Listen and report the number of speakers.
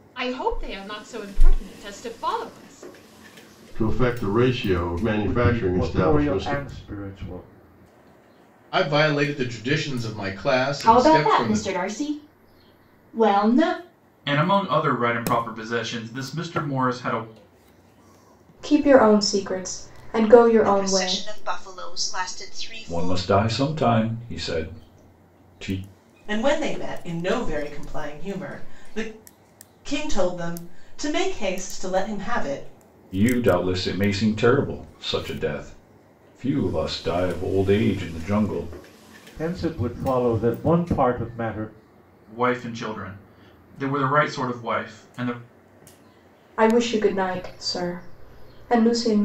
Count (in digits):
10